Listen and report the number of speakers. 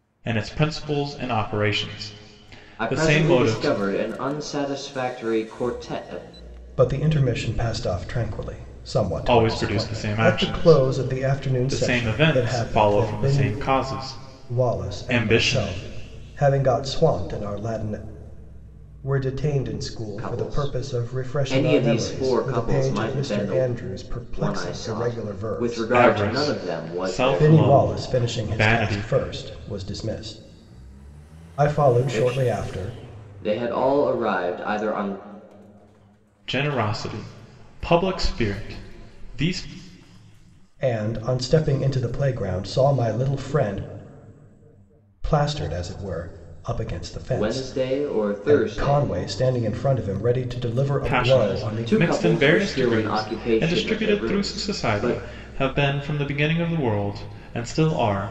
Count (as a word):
three